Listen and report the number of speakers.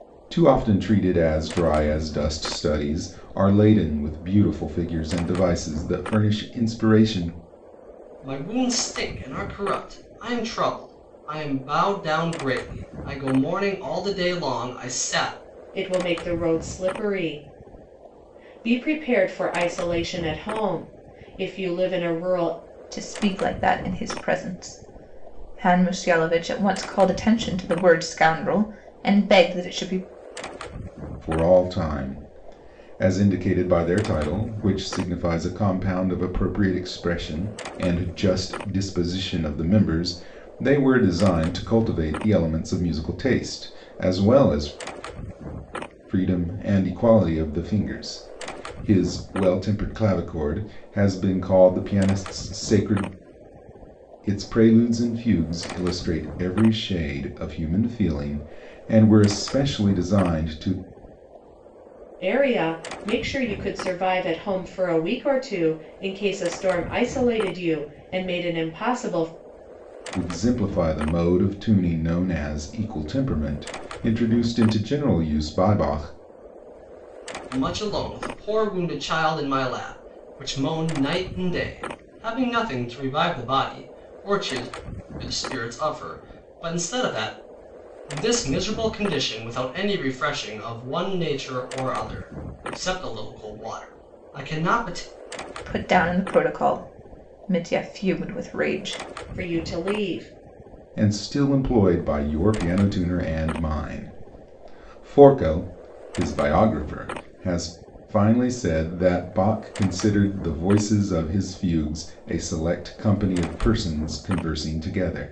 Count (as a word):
four